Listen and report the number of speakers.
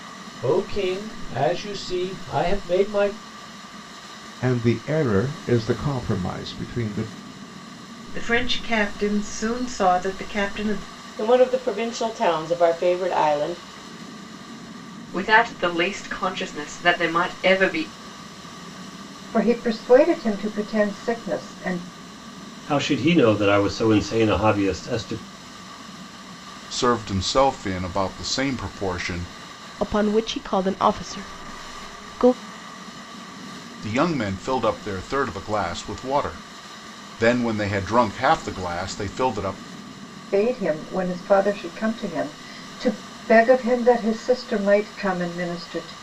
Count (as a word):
nine